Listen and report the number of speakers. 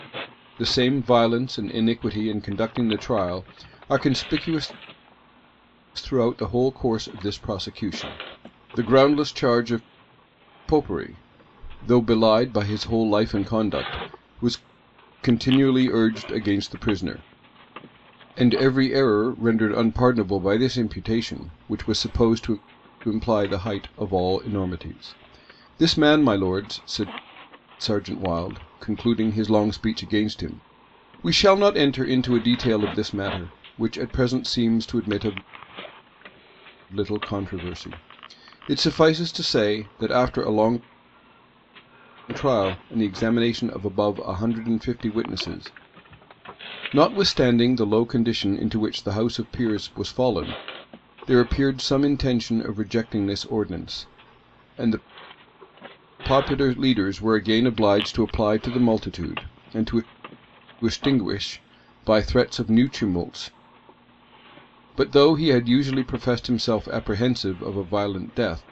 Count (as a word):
one